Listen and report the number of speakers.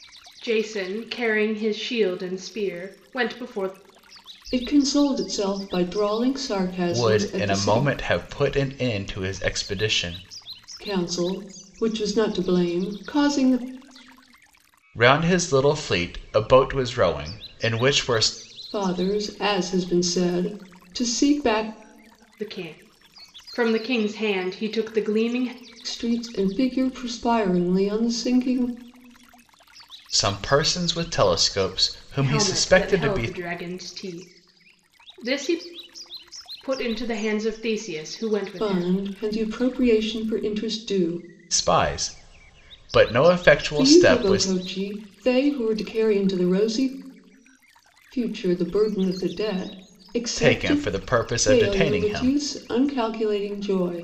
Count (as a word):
three